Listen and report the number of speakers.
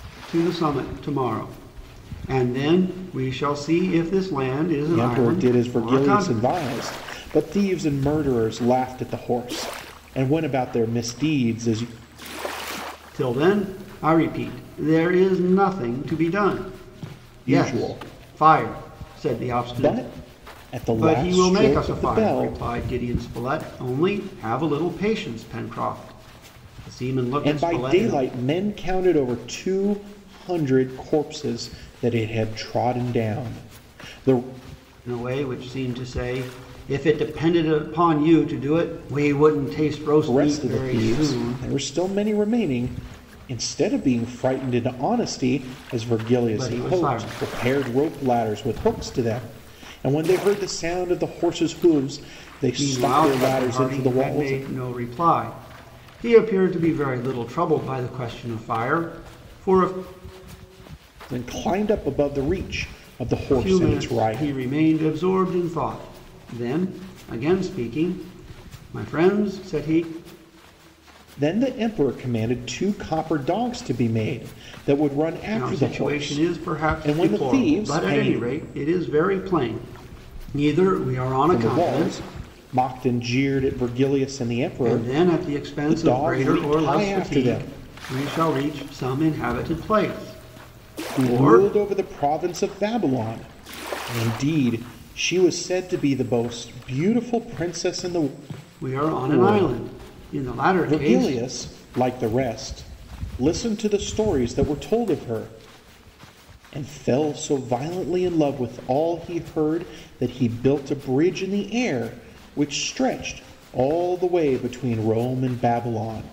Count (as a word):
two